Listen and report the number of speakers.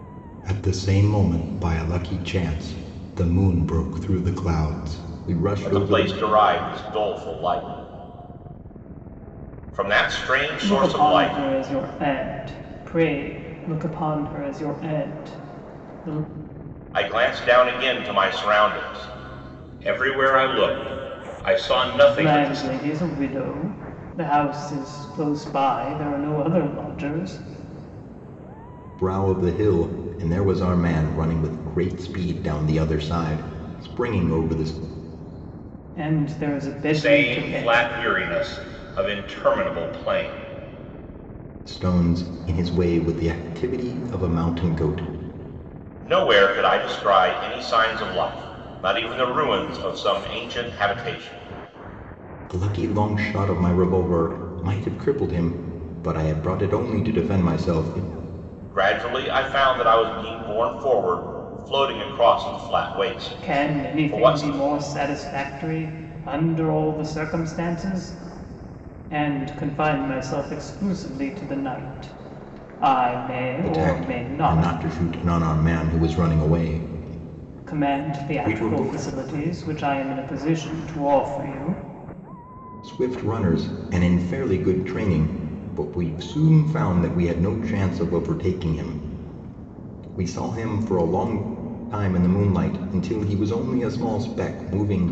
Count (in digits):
3